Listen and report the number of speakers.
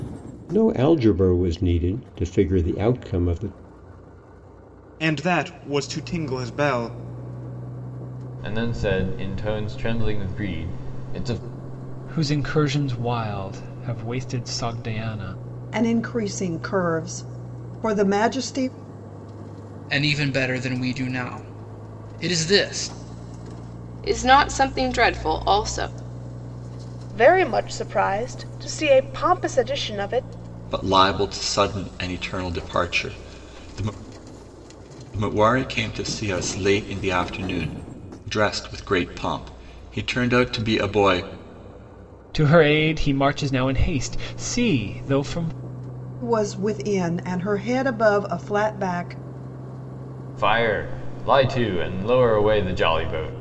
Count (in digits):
9